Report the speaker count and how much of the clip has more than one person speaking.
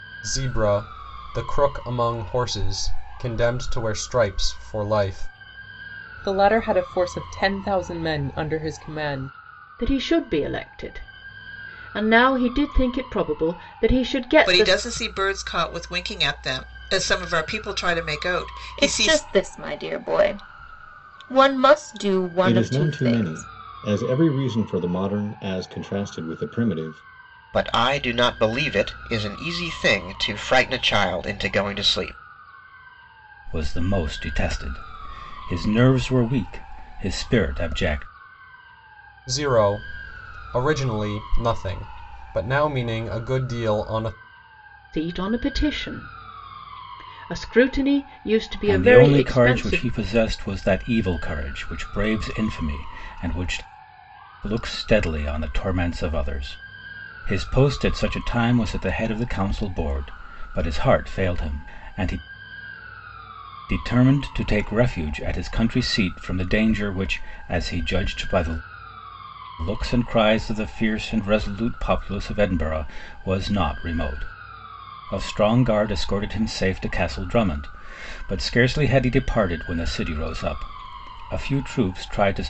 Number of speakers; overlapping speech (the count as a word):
eight, about 4%